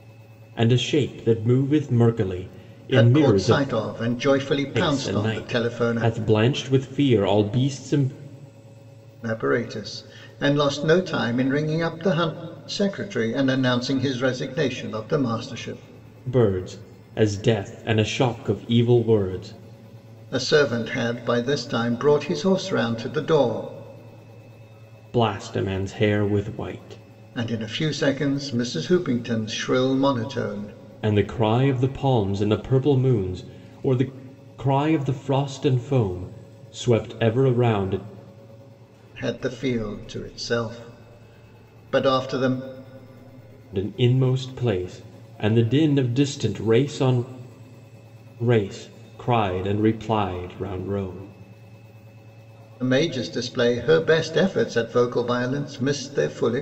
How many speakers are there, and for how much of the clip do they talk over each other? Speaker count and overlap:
two, about 4%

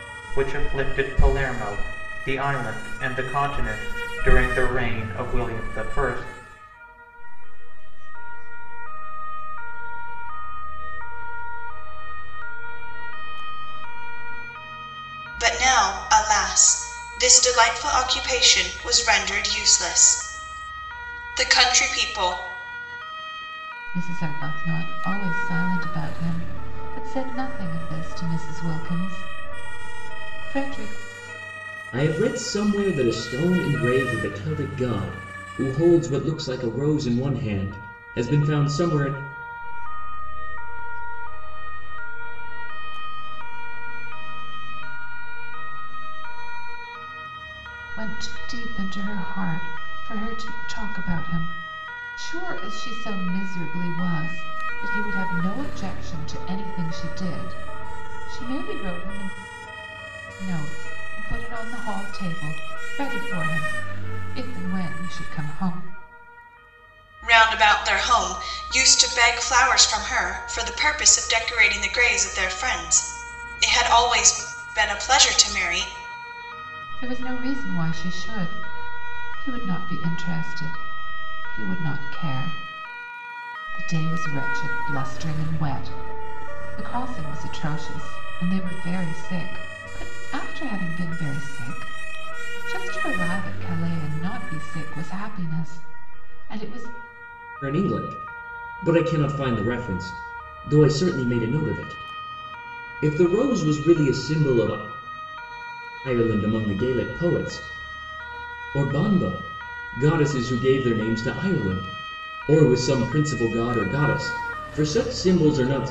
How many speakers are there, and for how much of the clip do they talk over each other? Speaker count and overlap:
five, no overlap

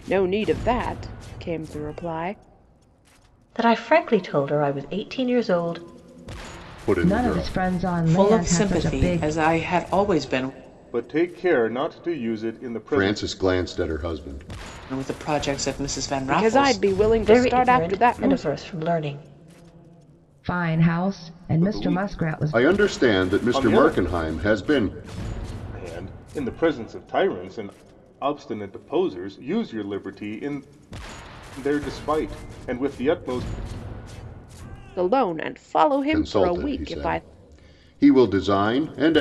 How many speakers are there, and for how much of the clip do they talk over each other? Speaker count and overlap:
six, about 20%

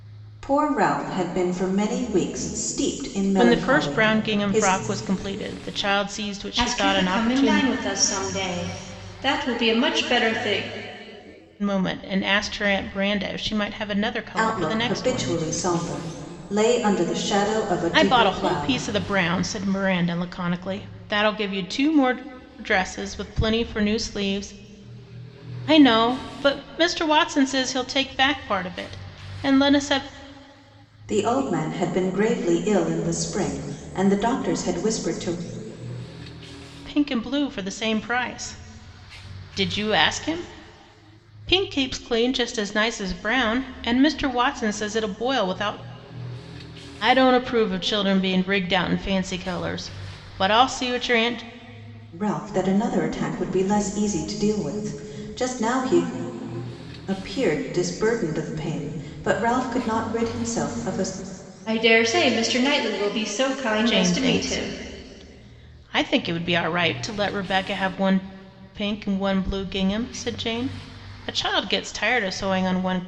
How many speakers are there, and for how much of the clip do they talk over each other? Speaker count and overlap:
three, about 8%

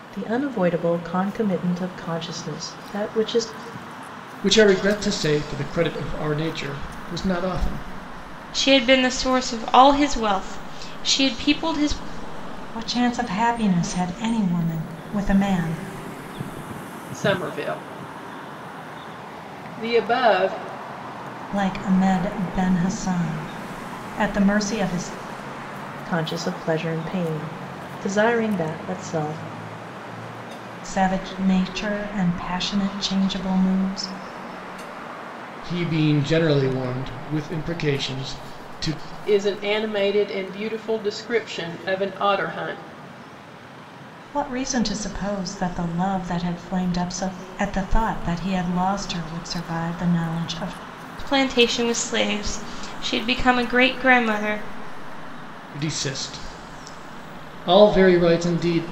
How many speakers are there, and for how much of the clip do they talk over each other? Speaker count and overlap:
five, no overlap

